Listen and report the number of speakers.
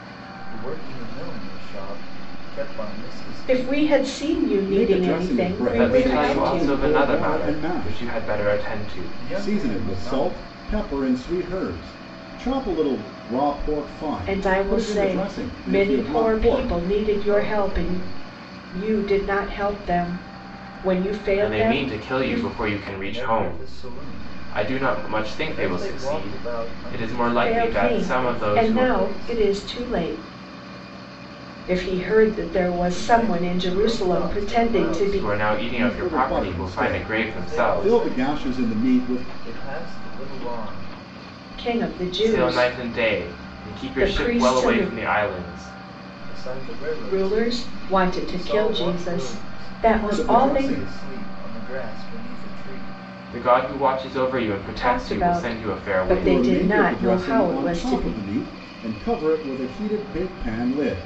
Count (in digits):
4